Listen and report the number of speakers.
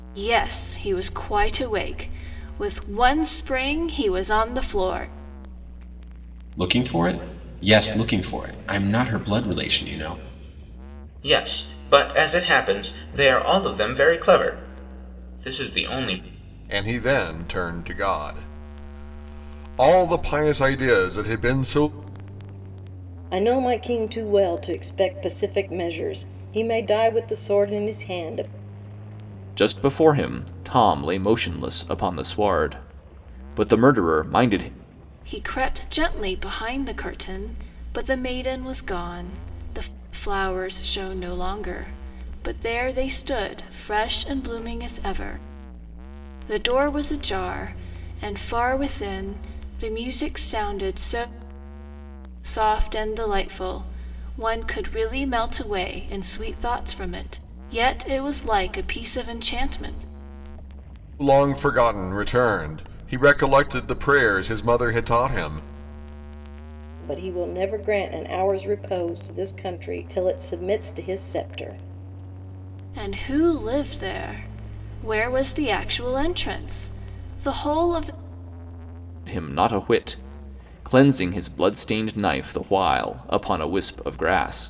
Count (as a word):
six